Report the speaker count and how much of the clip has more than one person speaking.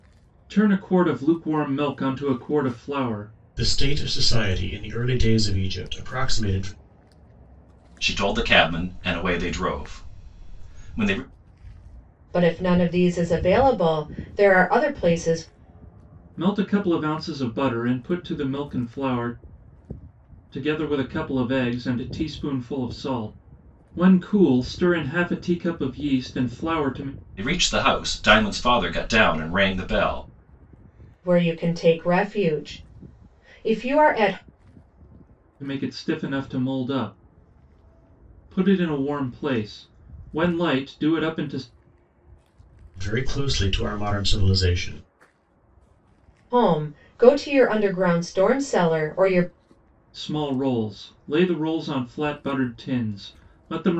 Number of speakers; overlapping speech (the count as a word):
four, no overlap